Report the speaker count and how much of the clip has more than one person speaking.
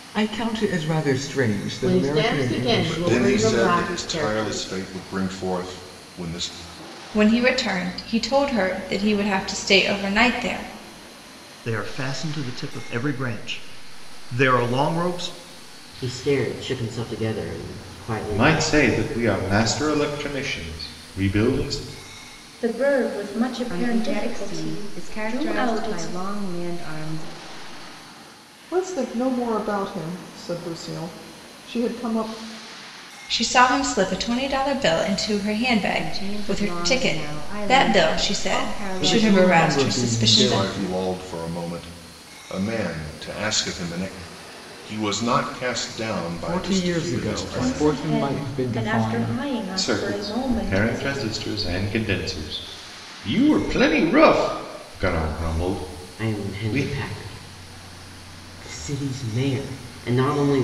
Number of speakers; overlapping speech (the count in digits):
10, about 27%